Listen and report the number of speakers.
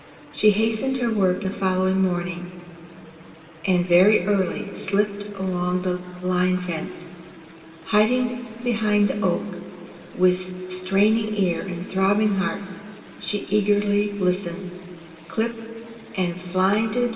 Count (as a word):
one